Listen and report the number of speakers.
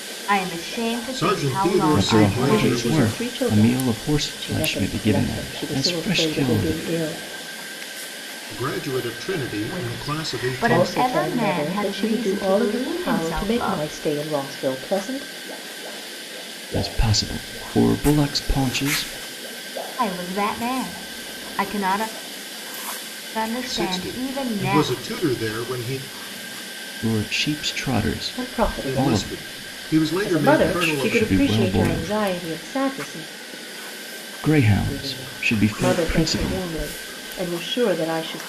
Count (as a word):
four